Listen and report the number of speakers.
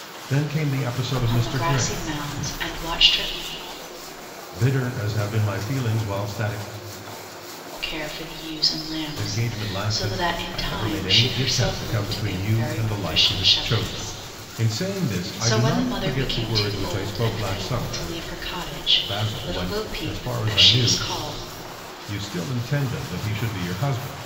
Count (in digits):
2